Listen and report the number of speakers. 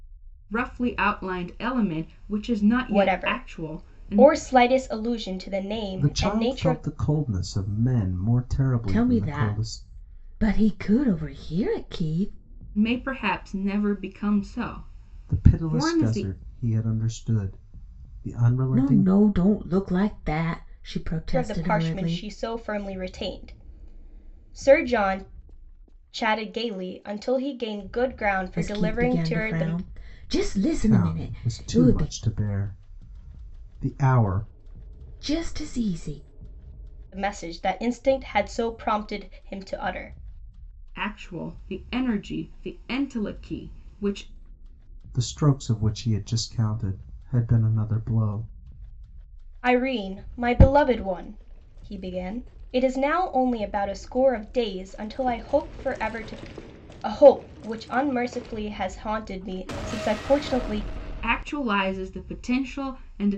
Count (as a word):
four